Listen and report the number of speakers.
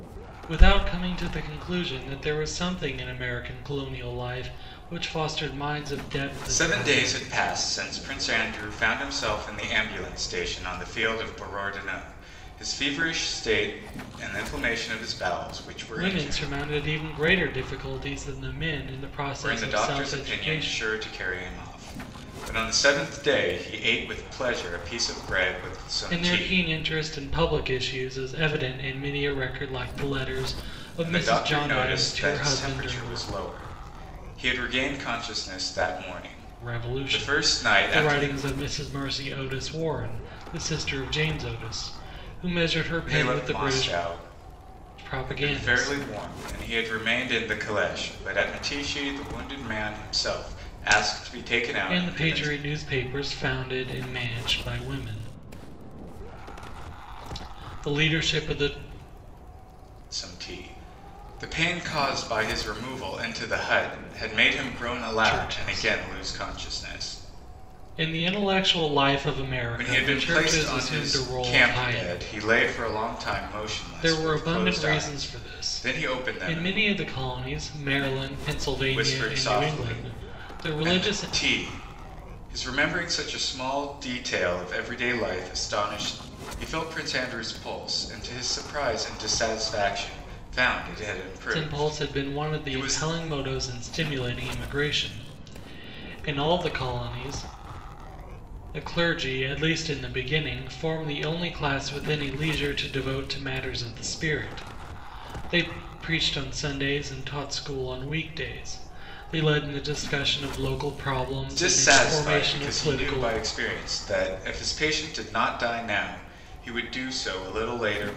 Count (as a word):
two